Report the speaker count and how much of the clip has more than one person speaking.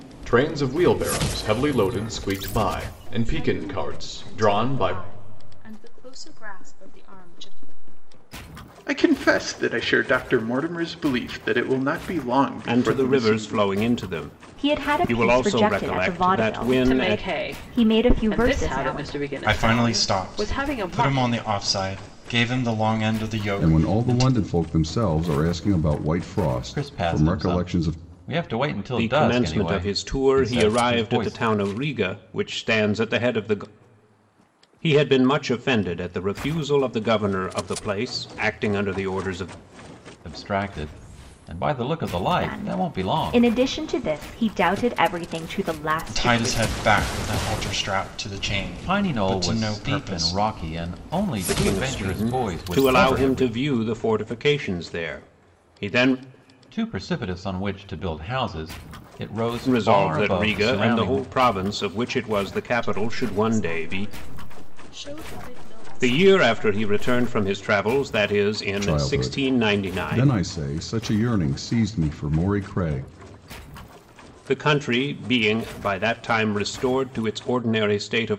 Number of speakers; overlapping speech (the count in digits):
9, about 34%